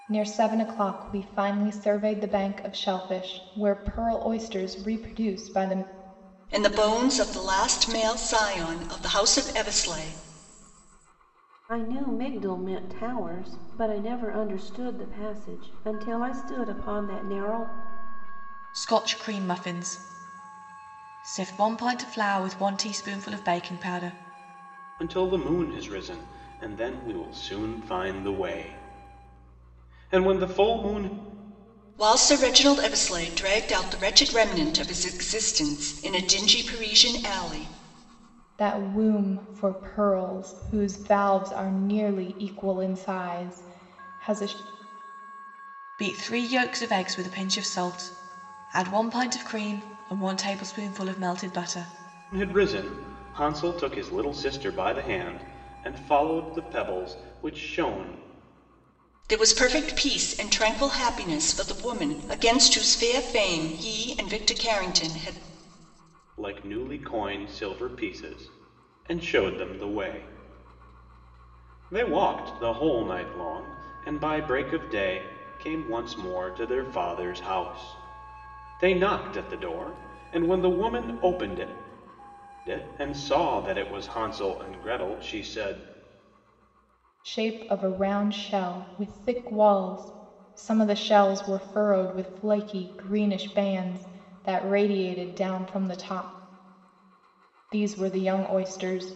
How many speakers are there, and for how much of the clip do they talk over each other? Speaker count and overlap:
five, no overlap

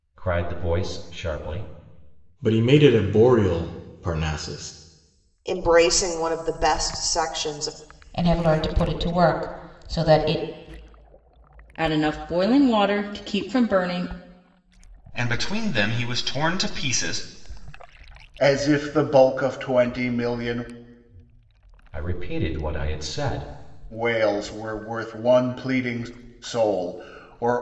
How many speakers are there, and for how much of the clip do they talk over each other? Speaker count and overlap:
seven, no overlap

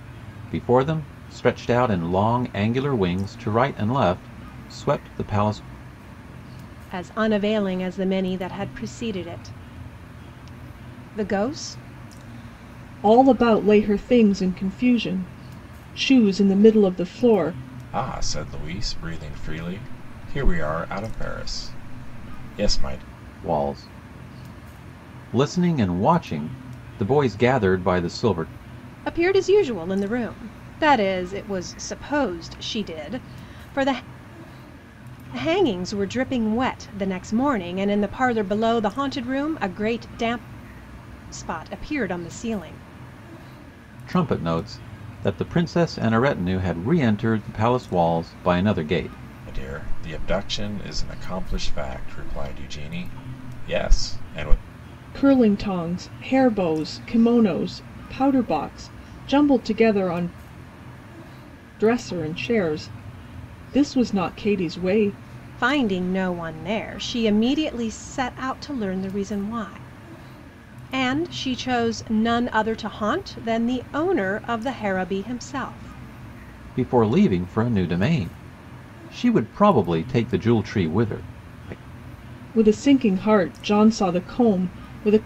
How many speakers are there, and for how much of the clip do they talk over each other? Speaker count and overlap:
four, no overlap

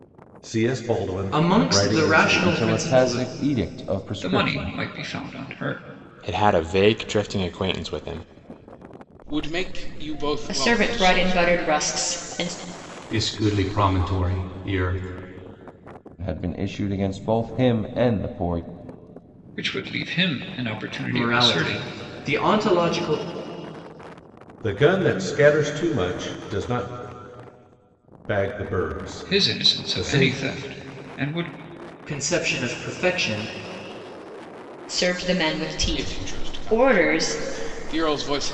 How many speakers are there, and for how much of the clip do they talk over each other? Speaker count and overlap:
eight, about 19%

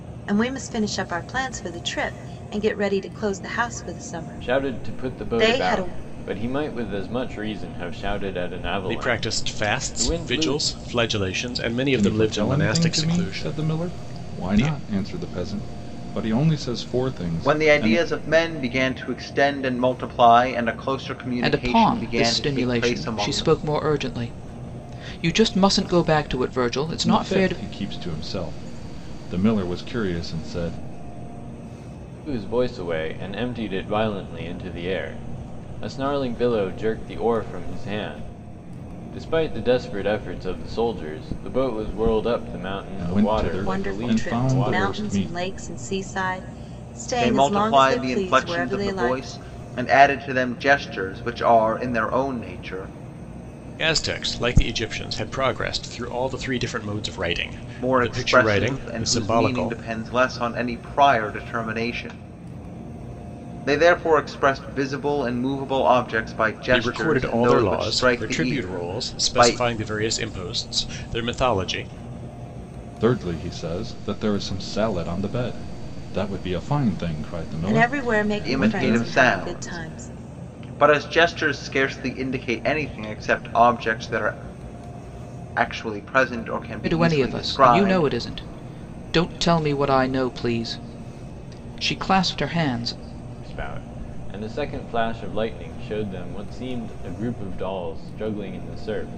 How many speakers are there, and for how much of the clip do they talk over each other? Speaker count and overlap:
six, about 23%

